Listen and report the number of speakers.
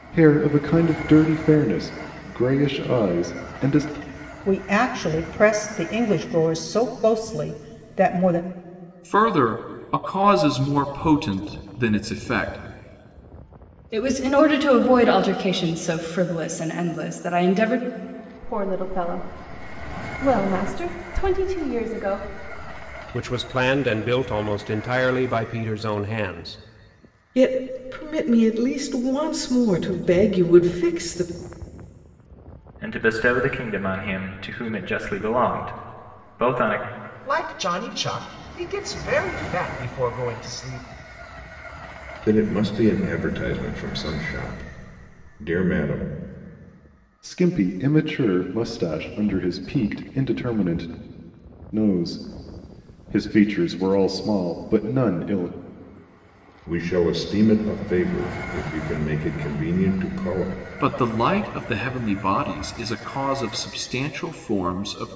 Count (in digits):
10